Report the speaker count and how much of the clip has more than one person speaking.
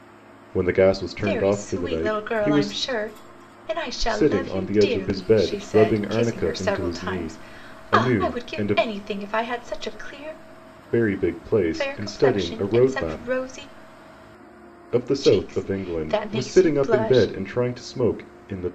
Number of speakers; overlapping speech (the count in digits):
2, about 54%